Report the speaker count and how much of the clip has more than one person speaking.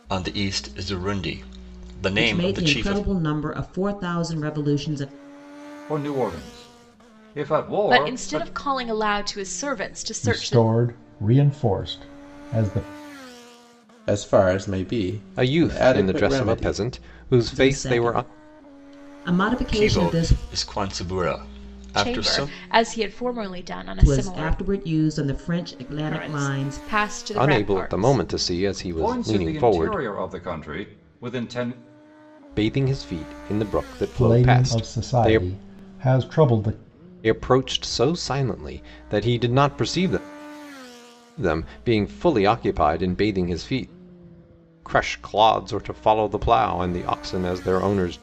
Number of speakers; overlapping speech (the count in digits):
7, about 22%